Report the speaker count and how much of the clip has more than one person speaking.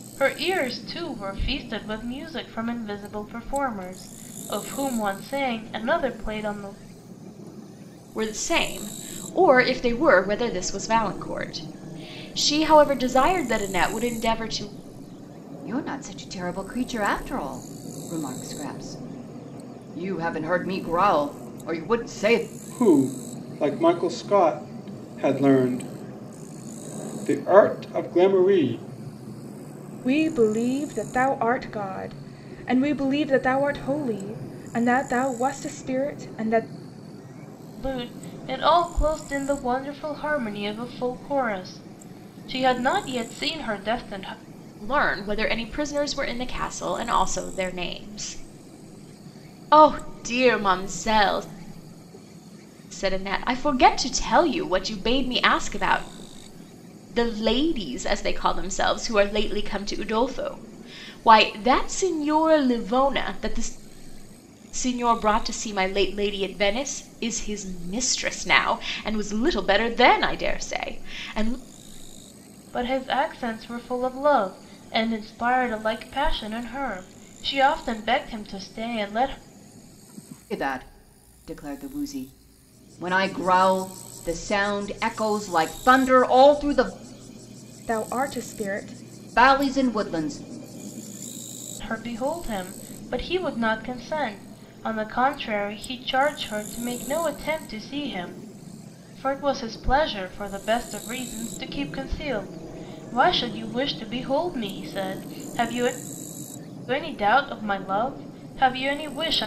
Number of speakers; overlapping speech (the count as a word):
five, no overlap